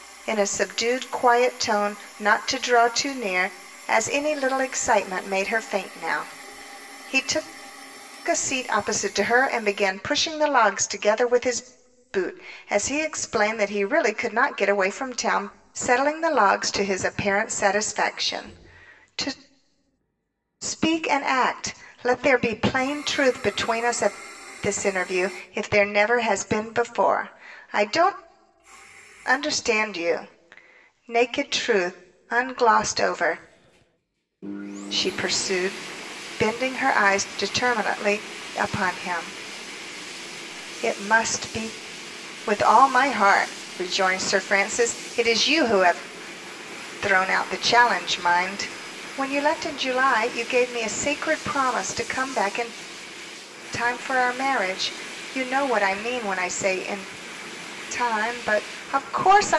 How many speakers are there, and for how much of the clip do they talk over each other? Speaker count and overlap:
one, no overlap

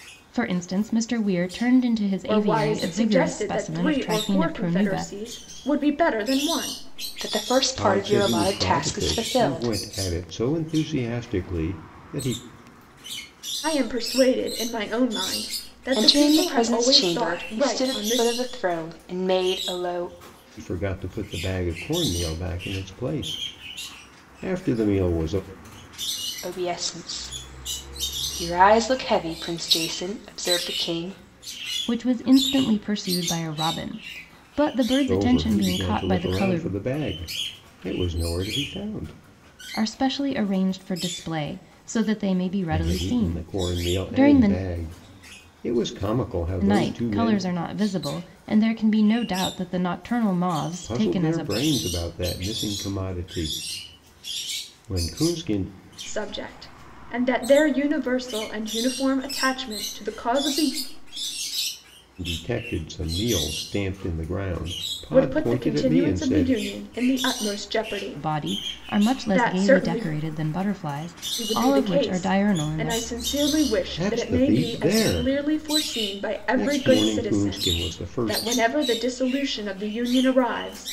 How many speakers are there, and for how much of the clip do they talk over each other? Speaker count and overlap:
four, about 28%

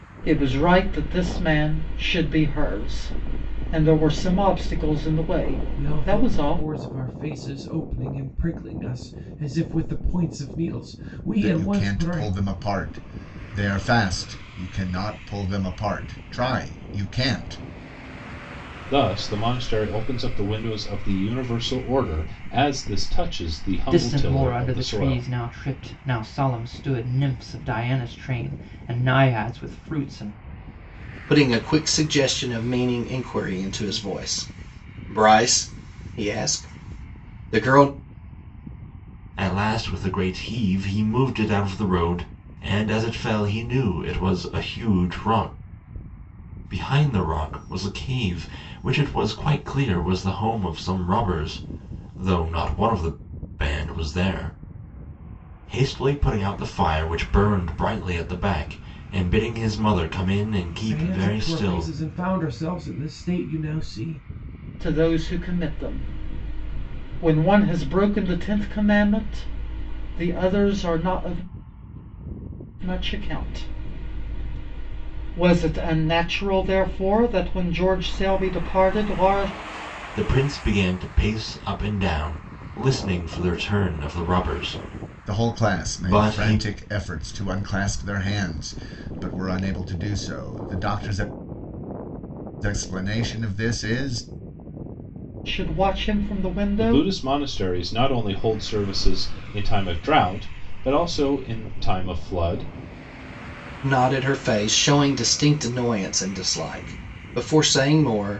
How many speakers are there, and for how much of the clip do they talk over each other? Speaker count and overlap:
seven, about 6%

